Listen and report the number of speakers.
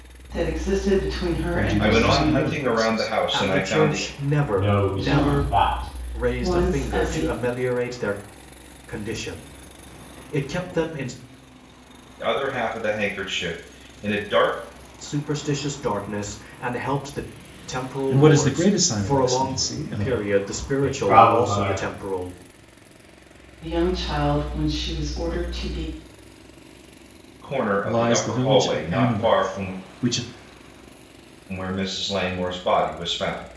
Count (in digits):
5